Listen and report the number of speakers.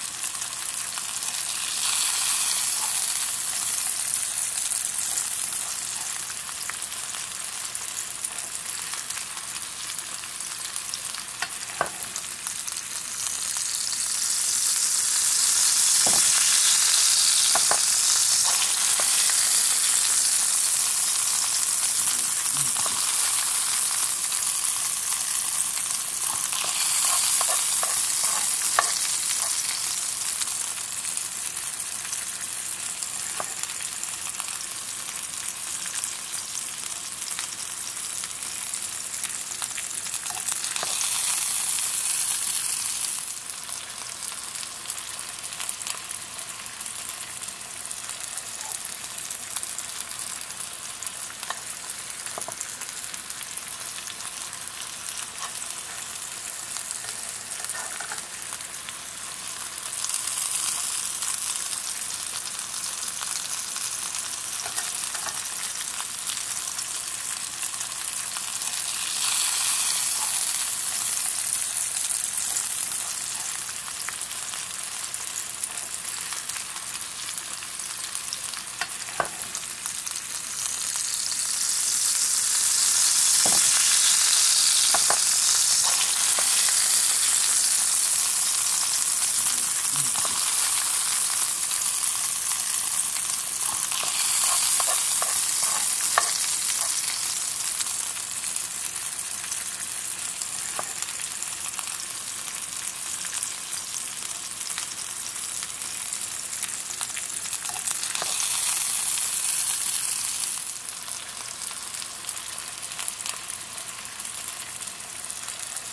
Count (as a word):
zero